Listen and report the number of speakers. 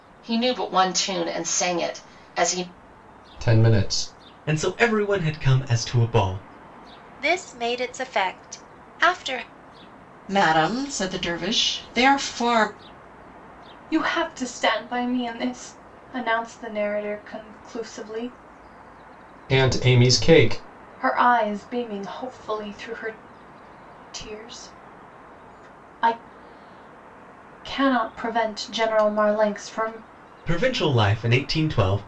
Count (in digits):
6